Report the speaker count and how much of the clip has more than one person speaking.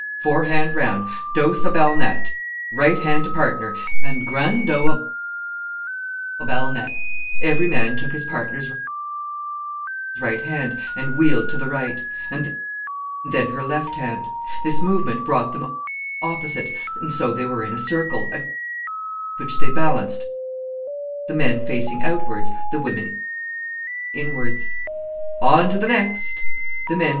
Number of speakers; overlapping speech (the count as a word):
one, no overlap